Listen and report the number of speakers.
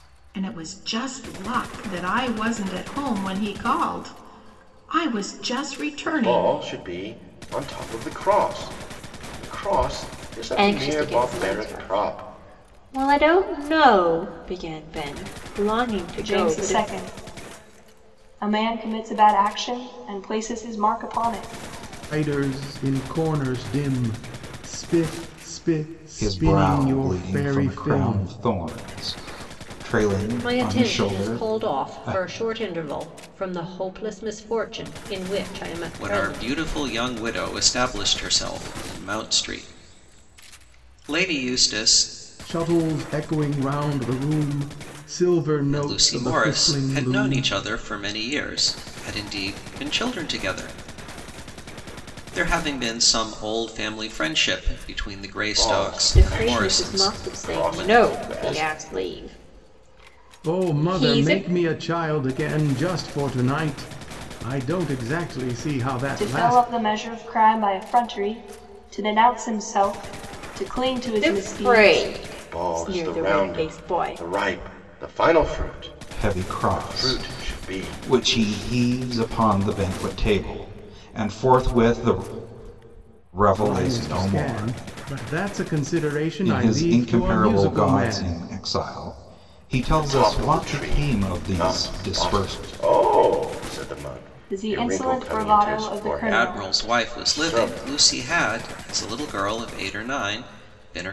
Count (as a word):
eight